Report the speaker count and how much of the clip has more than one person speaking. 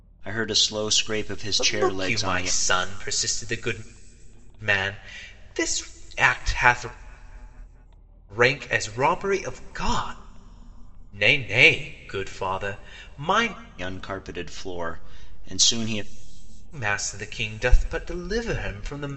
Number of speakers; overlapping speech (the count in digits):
2, about 5%